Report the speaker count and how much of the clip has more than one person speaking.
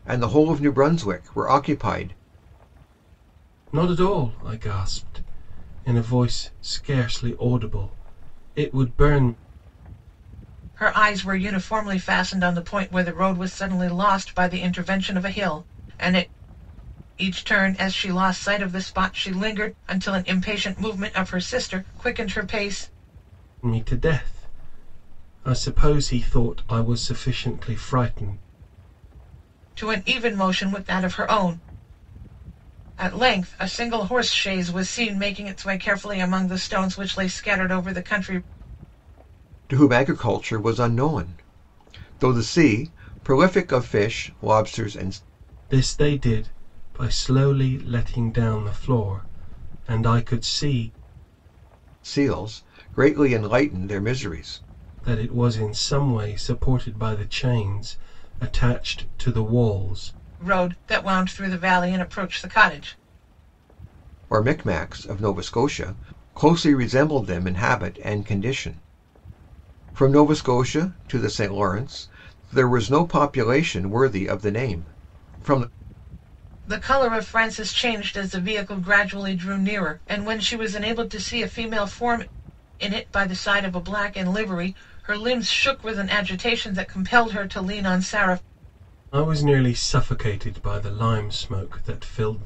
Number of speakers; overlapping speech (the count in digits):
3, no overlap